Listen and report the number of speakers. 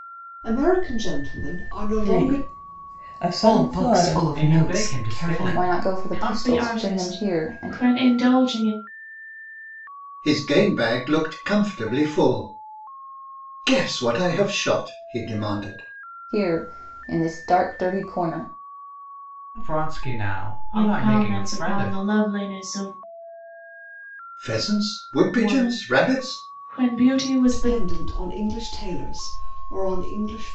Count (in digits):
7